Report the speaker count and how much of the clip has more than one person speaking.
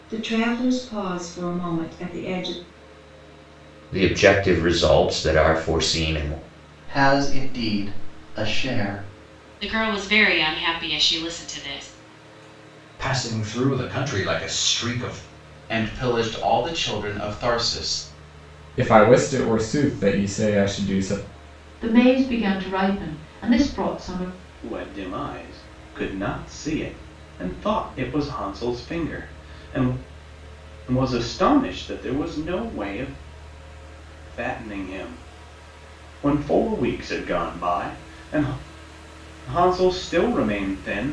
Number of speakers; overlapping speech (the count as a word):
nine, no overlap